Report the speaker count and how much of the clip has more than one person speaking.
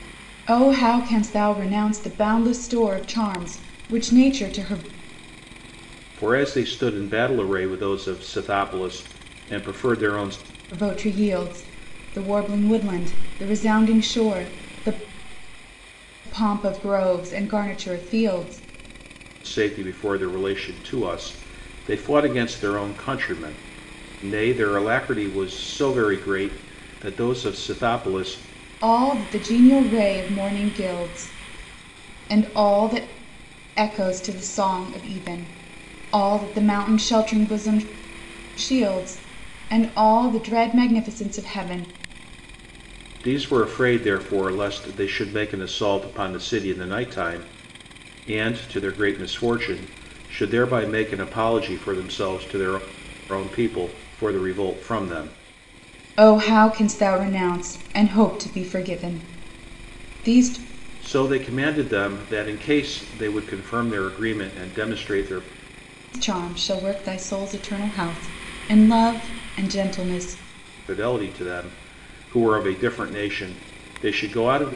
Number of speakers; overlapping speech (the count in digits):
2, no overlap